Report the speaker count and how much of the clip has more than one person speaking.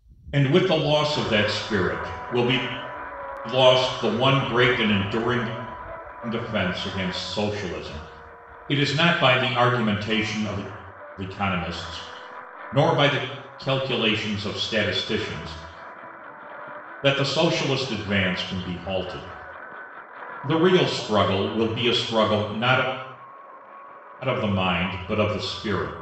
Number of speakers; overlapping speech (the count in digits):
1, no overlap